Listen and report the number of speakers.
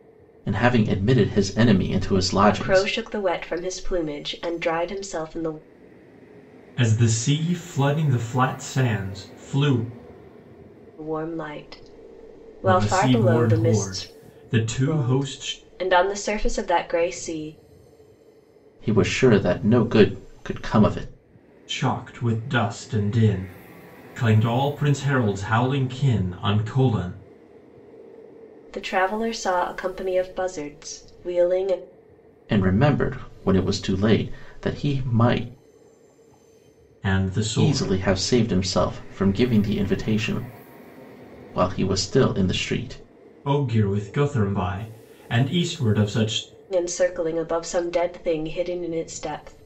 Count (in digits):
3